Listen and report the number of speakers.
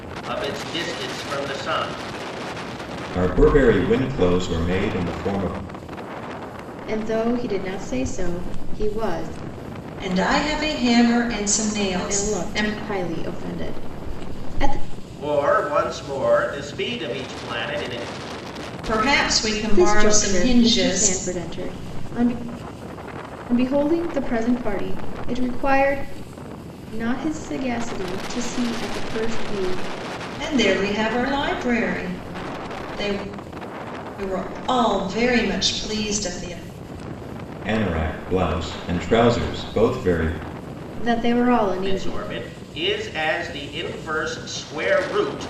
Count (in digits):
4